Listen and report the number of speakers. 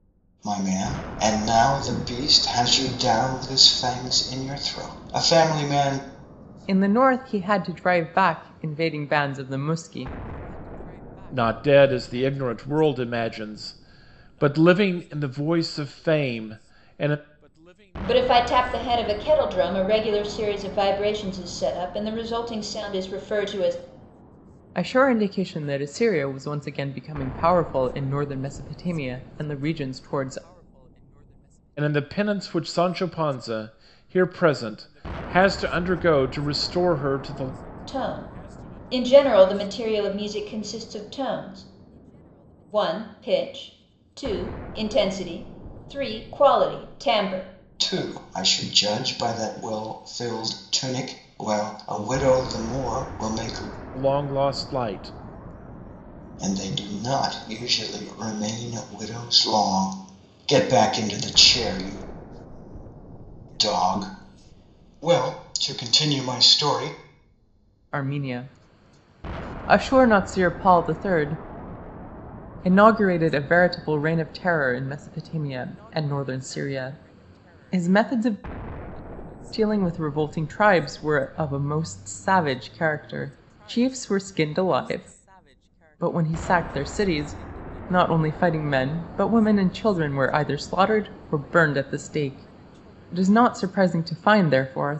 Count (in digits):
4